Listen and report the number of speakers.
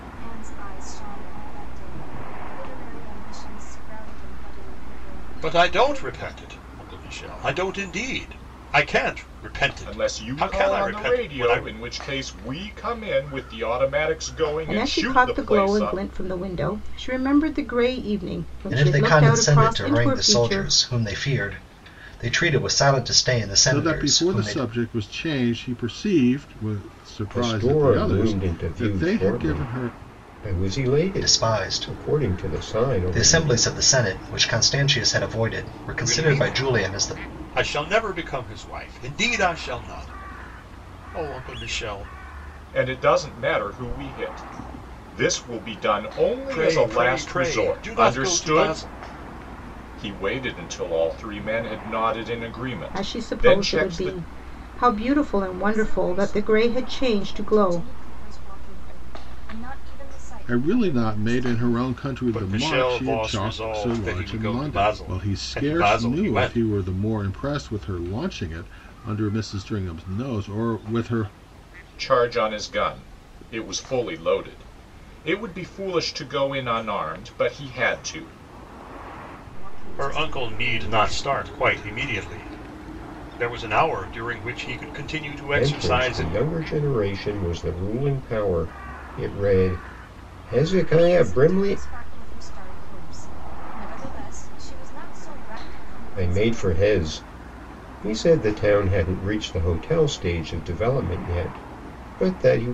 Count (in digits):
7